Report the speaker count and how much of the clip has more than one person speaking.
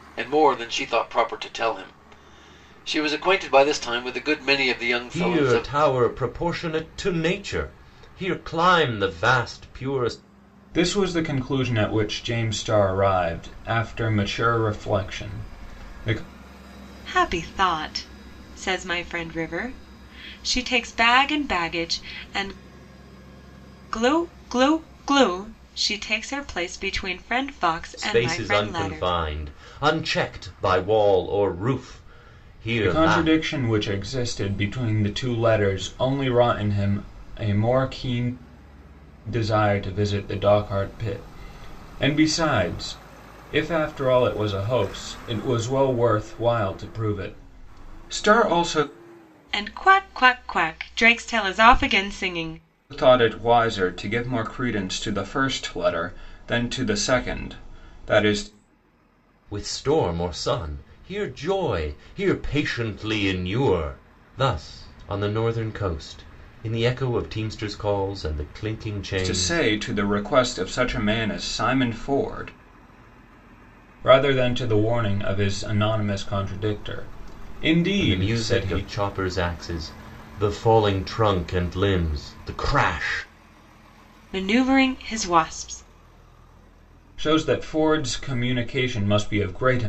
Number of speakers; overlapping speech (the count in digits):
4, about 4%